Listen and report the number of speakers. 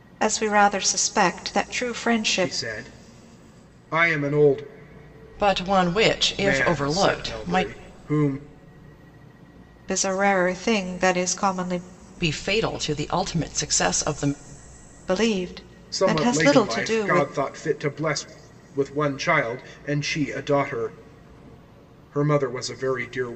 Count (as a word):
three